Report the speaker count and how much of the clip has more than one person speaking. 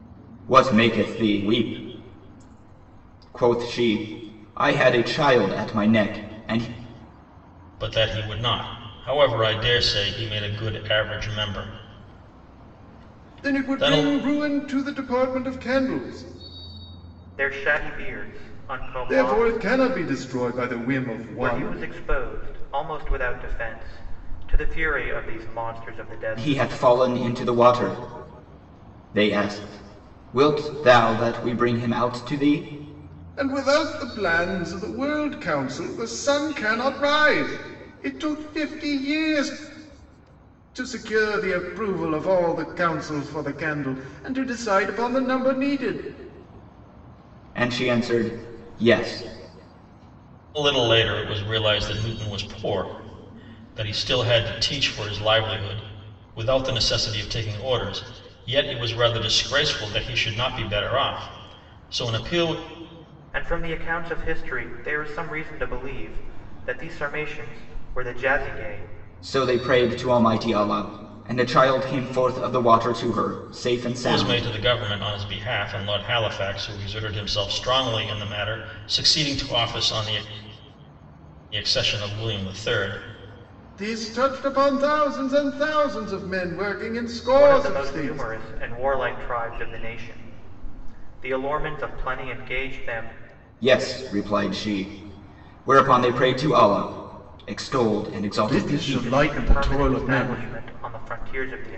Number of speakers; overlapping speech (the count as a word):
four, about 6%